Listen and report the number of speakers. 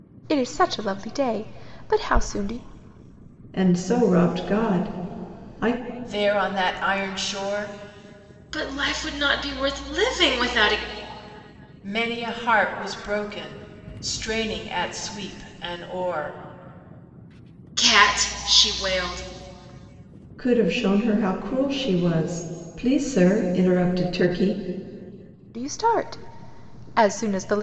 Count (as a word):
four